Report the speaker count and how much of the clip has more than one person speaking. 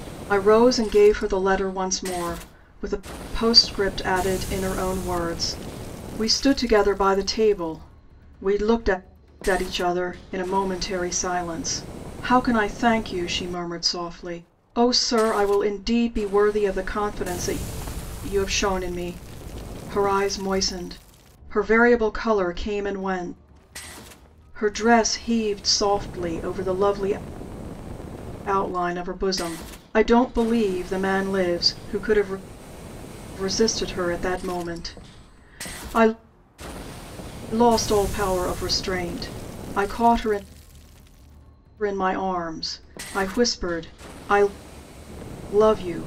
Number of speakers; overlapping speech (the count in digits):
1, no overlap